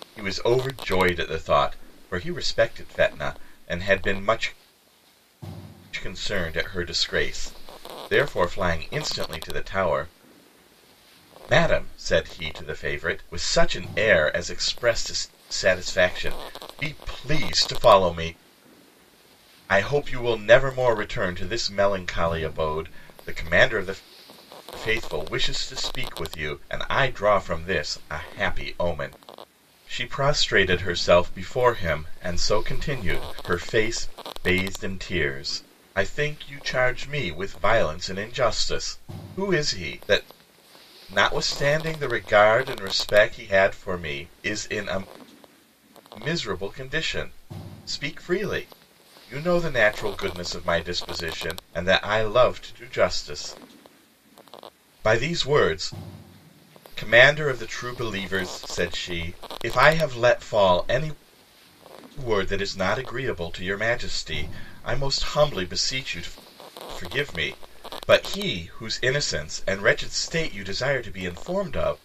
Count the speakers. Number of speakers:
1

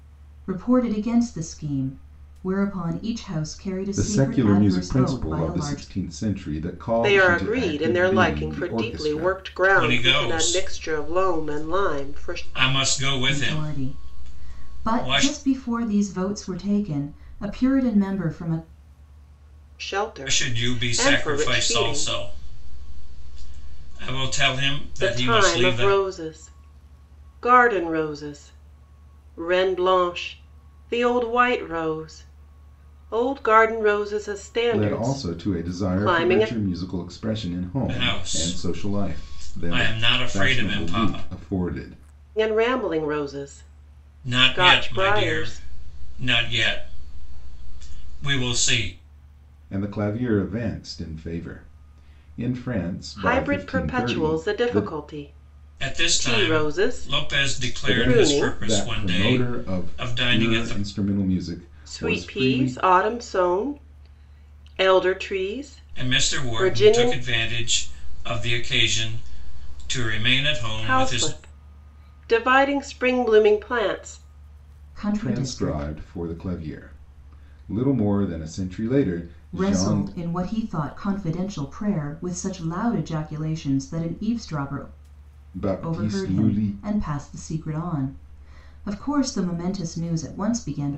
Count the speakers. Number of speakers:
4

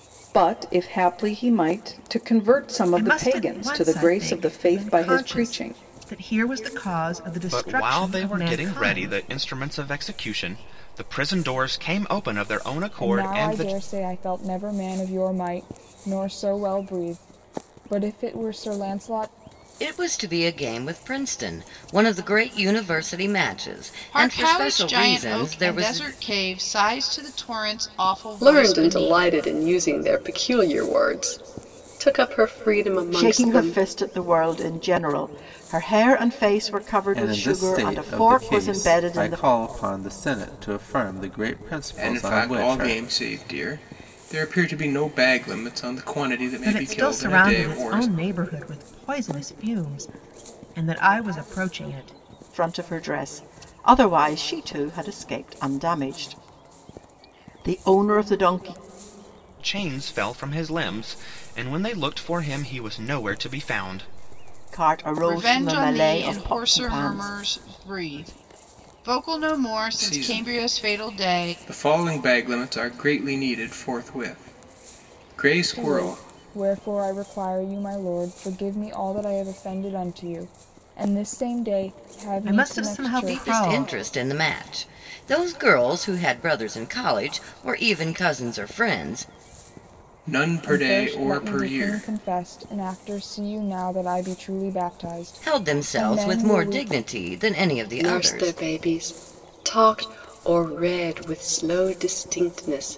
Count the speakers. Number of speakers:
10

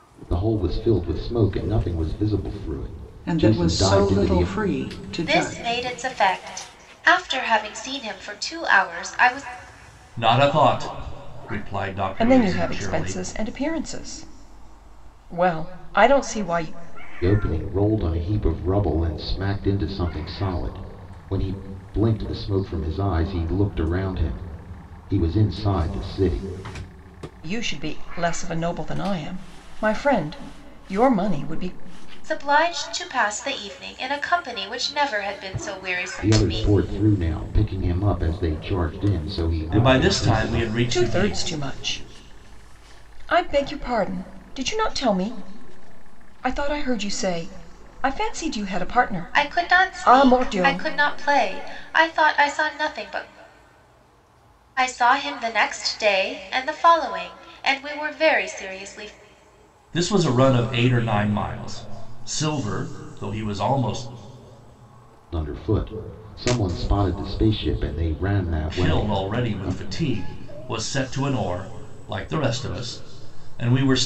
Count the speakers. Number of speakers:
5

